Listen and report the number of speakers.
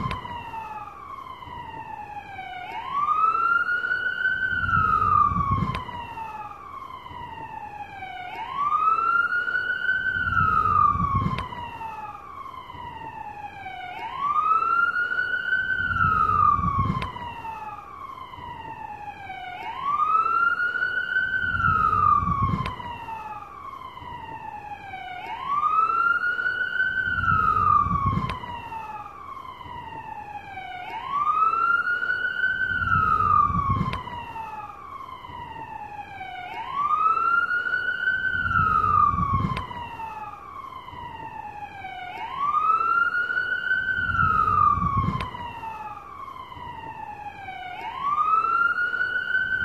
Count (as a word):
zero